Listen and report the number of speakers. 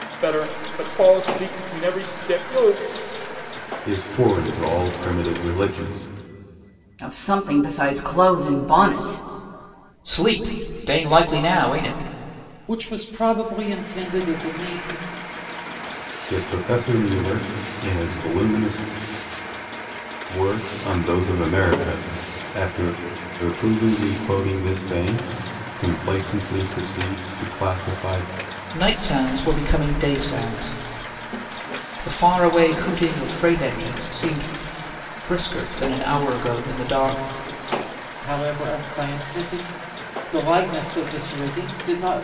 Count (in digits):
5